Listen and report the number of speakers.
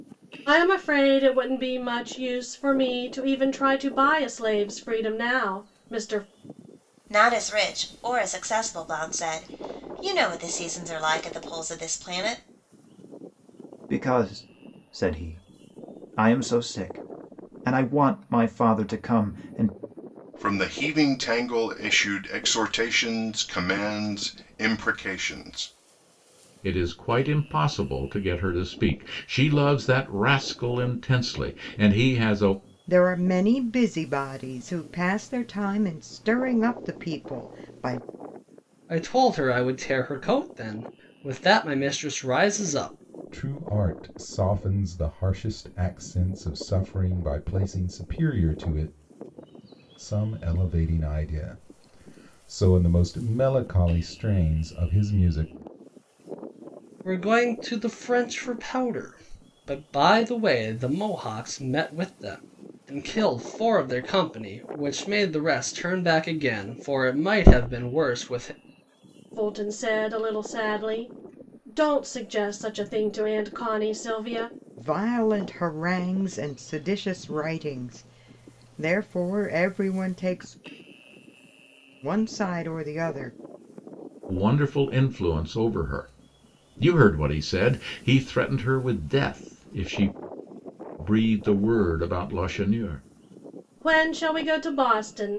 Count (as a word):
eight